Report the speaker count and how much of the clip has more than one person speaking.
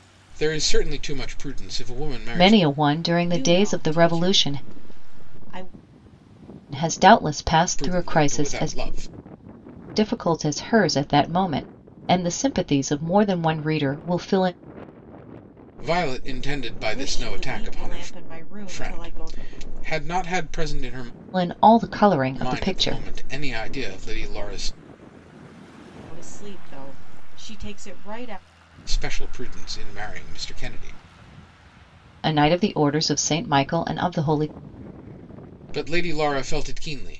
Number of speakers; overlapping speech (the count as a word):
three, about 15%